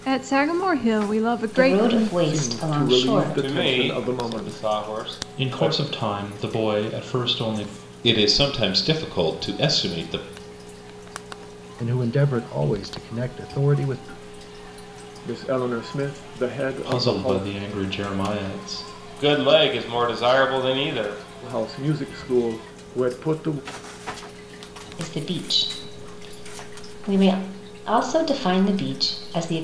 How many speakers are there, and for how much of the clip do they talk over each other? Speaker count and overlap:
7, about 14%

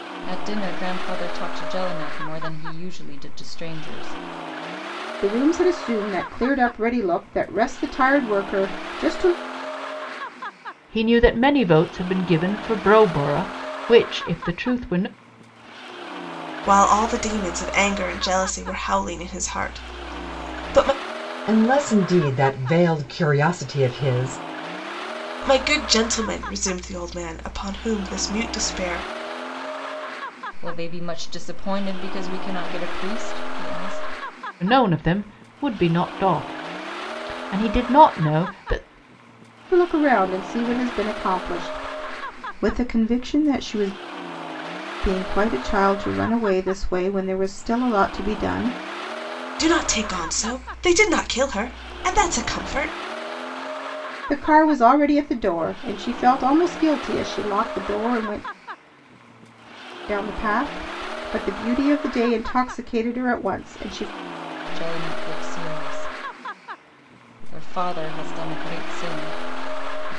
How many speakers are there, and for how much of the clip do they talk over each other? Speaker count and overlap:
5, no overlap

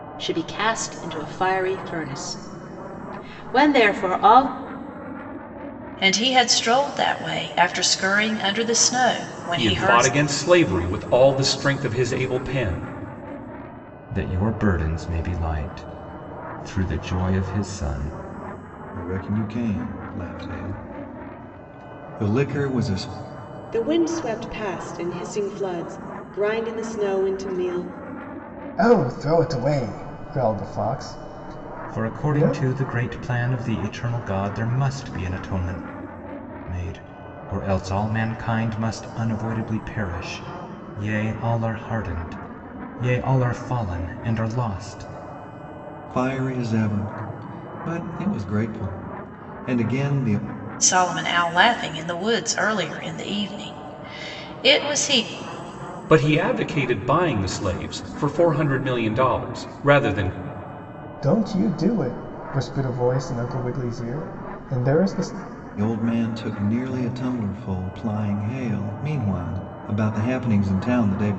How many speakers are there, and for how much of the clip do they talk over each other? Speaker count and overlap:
7, about 2%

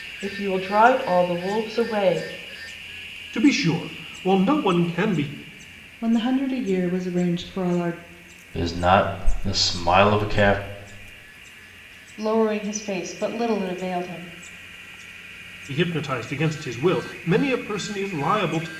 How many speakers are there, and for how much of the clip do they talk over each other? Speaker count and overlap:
5, no overlap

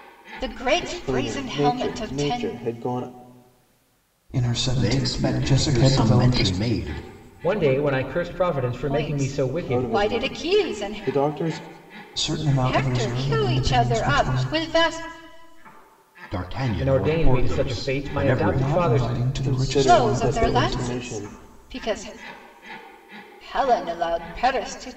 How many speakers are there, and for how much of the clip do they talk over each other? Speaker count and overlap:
5, about 48%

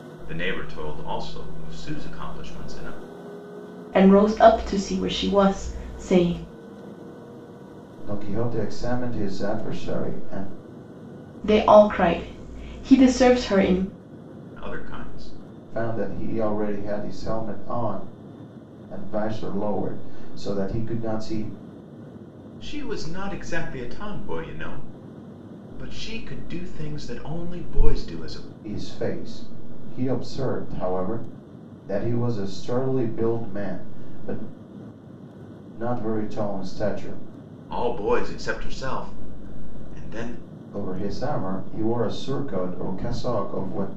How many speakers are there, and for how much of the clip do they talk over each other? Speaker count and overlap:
3, no overlap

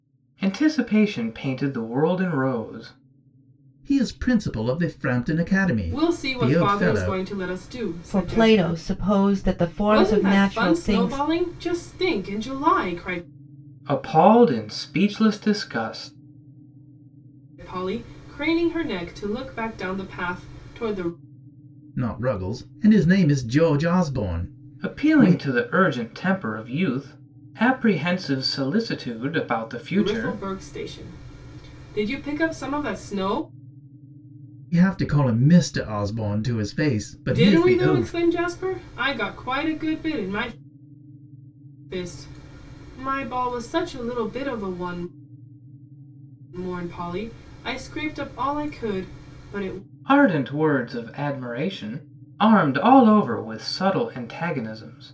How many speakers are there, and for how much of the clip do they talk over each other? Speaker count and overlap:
4, about 10%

